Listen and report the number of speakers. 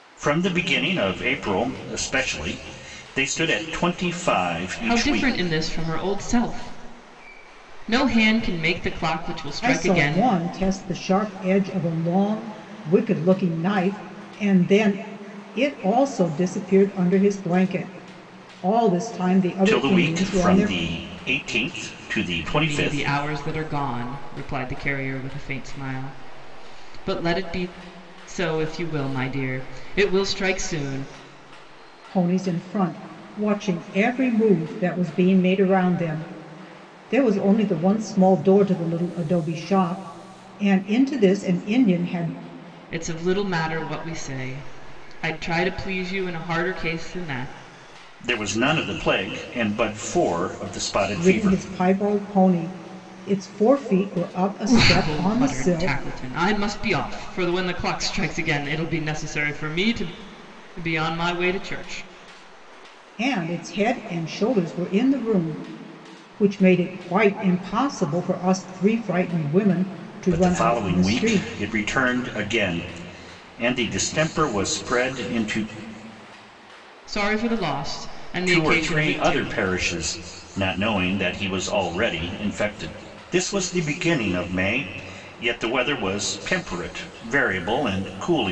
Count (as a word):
three